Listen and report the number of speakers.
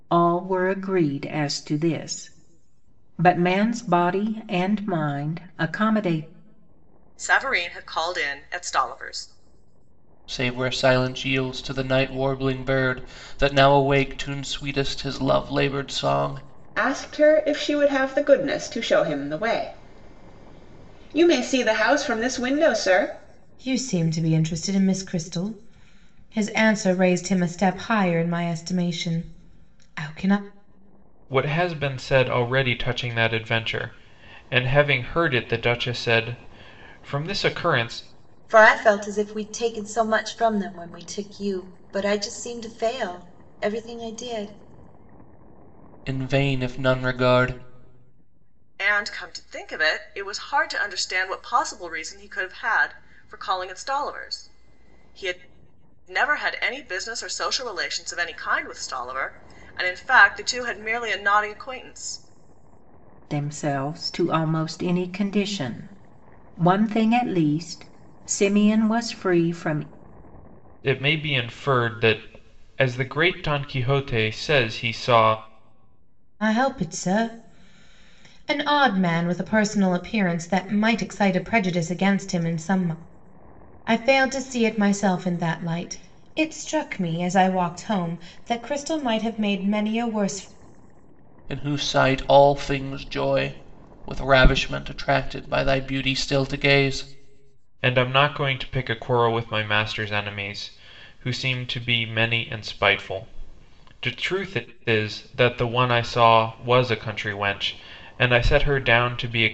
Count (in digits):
7